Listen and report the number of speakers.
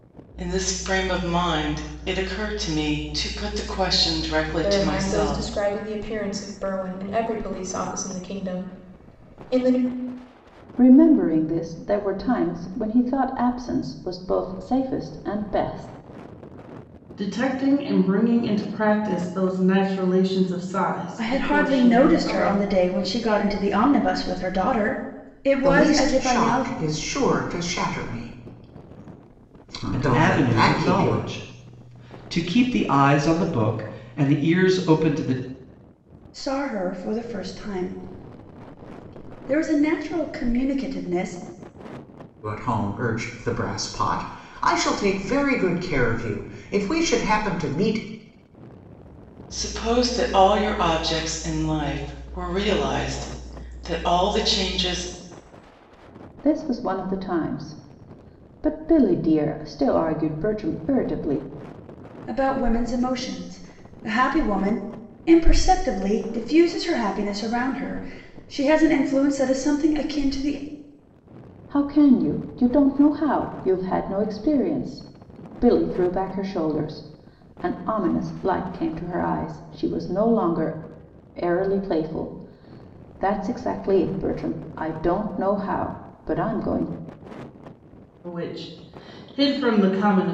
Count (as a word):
seven